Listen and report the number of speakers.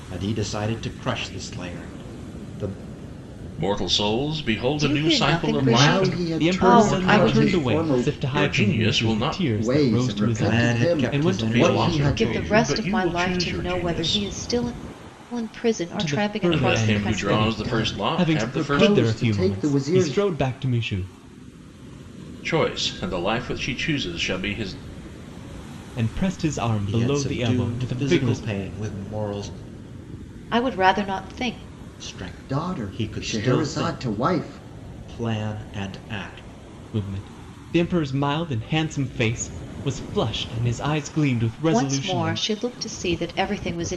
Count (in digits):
5